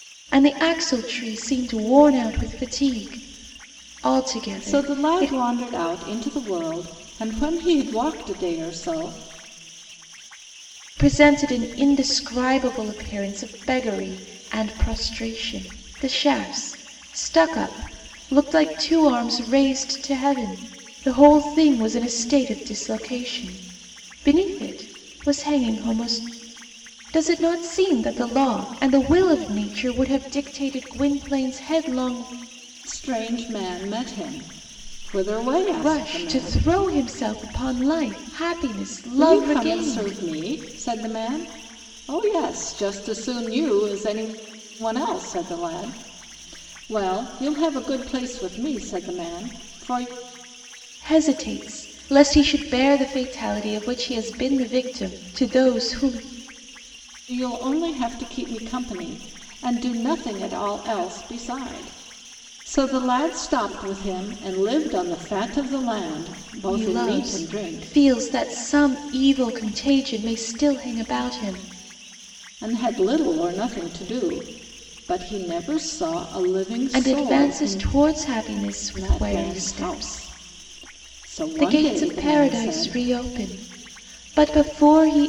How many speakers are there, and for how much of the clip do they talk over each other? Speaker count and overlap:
2, about 9%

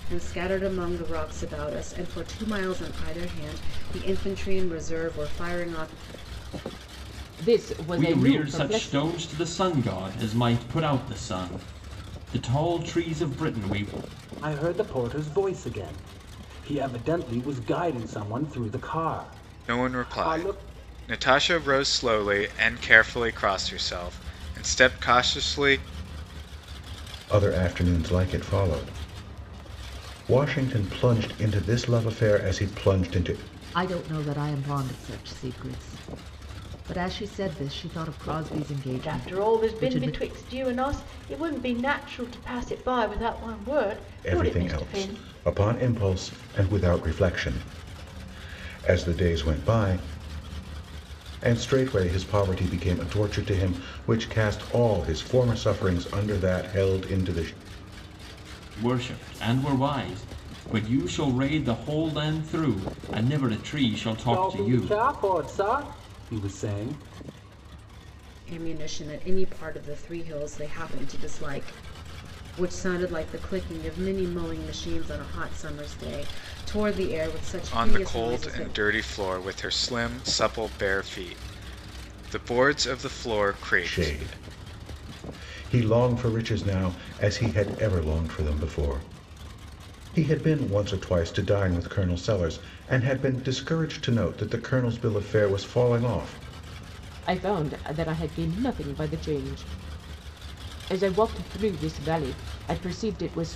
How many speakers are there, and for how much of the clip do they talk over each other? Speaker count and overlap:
8, about 6%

